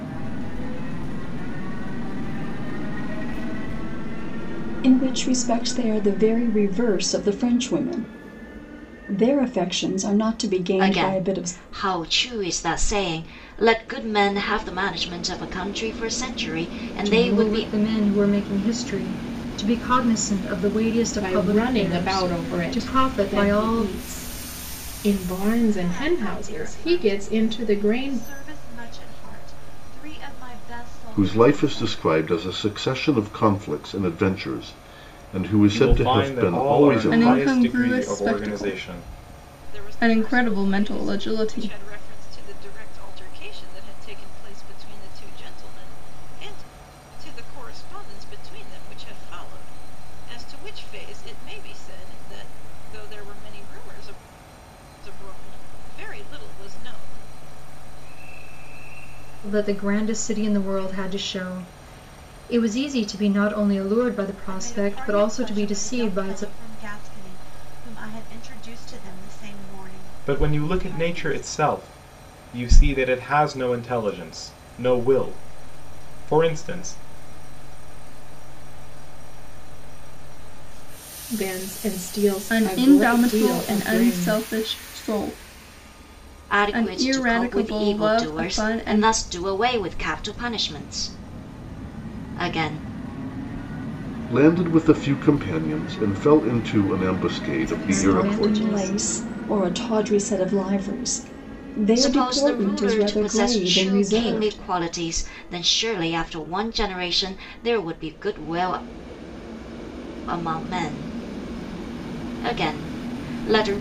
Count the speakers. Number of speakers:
10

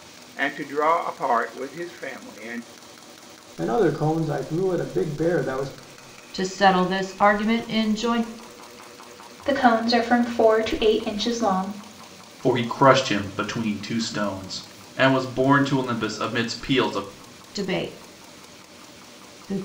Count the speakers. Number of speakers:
5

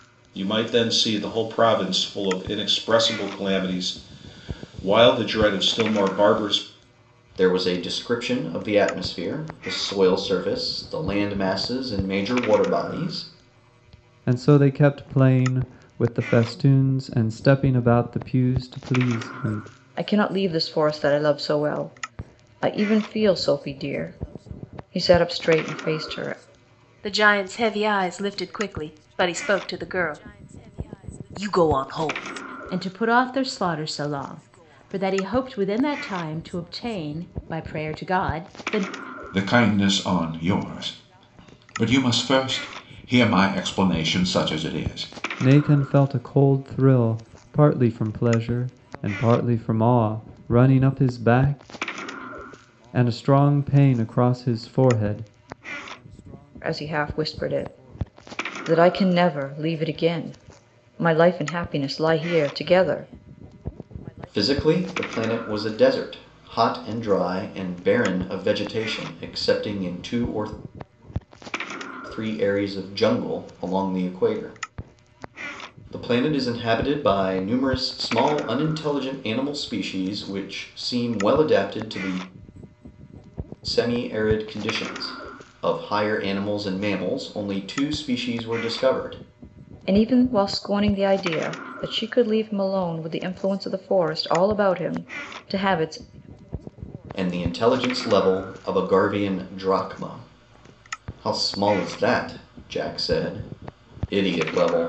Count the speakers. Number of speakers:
7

